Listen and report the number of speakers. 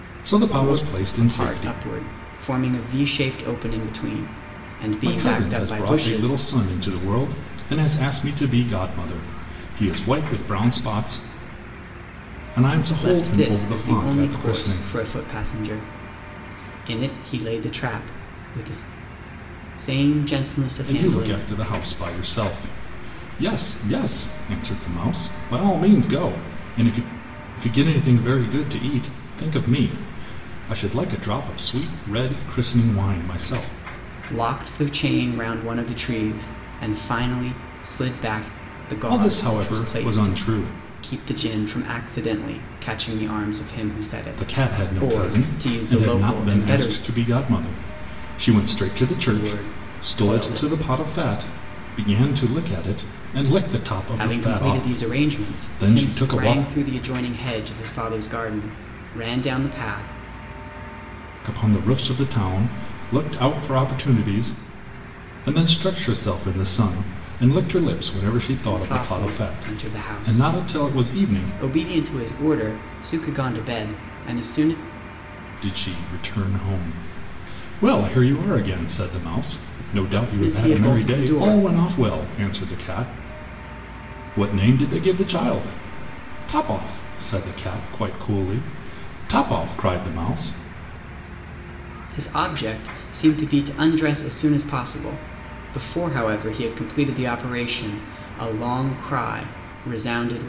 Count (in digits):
2